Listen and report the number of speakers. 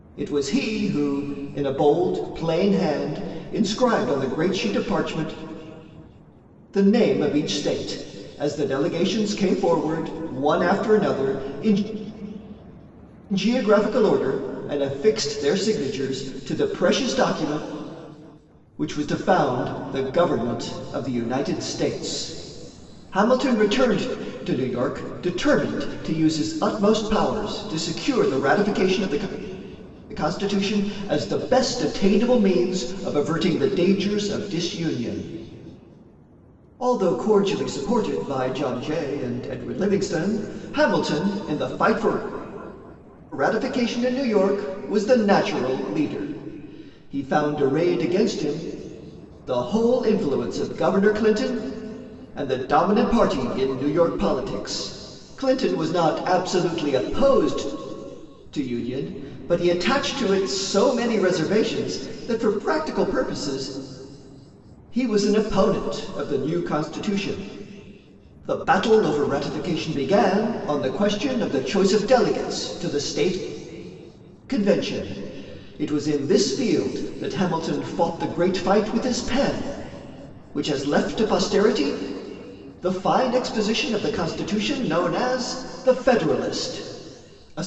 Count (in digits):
1